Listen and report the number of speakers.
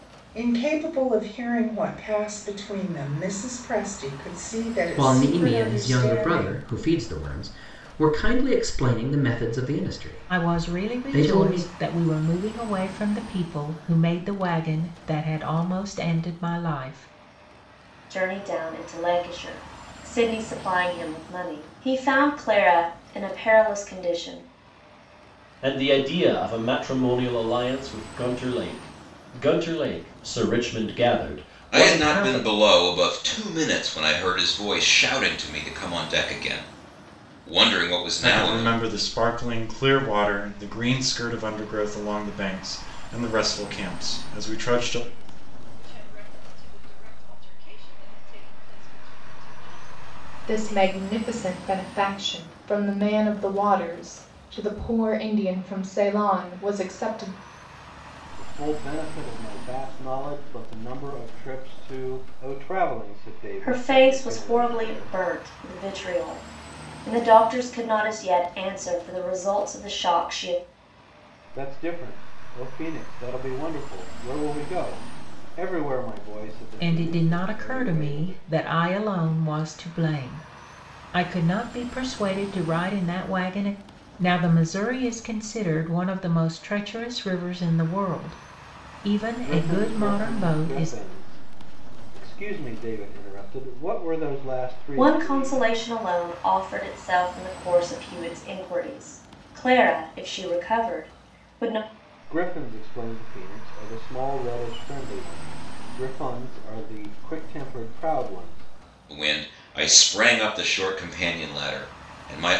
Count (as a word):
ten